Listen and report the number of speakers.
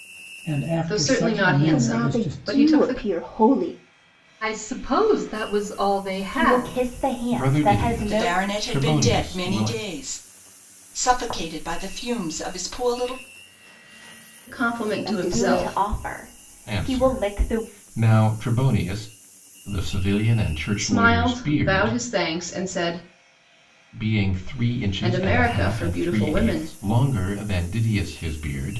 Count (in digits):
7